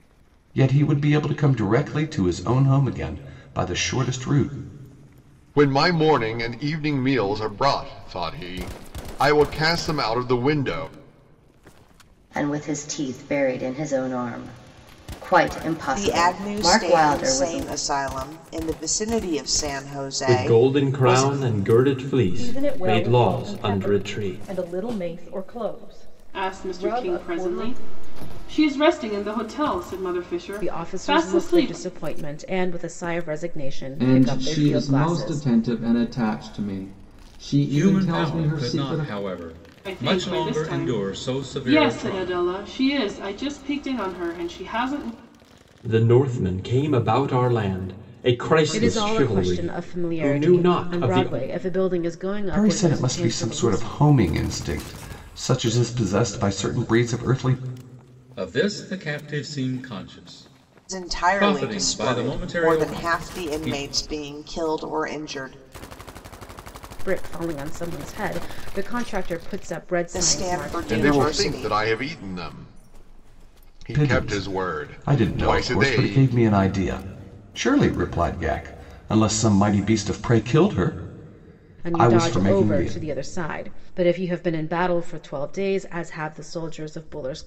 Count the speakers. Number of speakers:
10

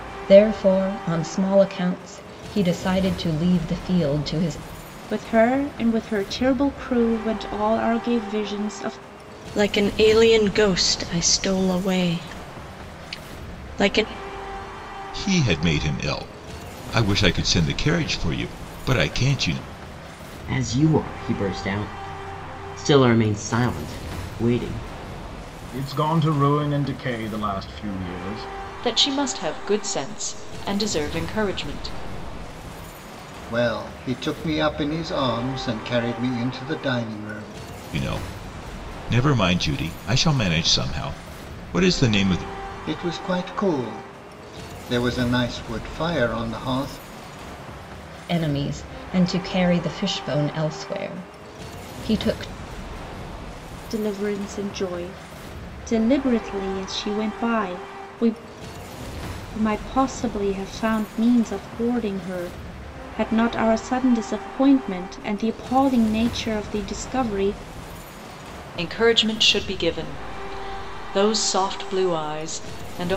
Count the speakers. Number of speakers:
8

